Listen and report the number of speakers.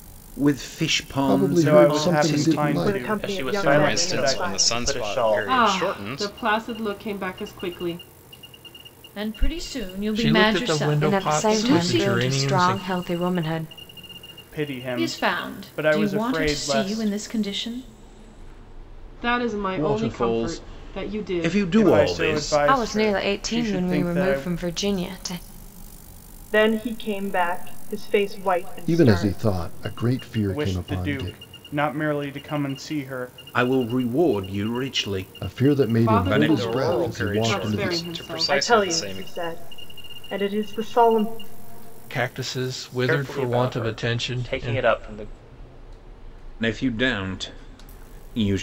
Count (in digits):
10